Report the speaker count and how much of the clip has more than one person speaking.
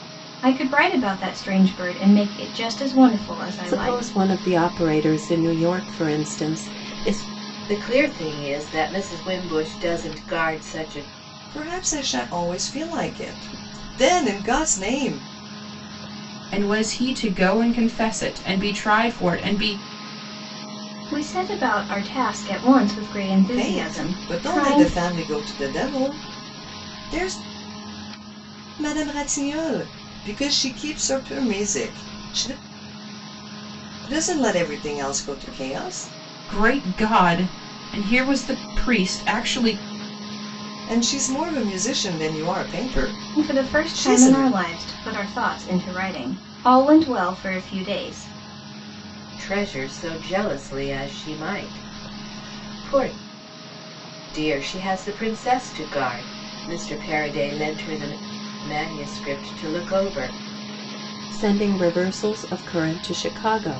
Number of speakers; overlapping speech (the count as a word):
five, about 5%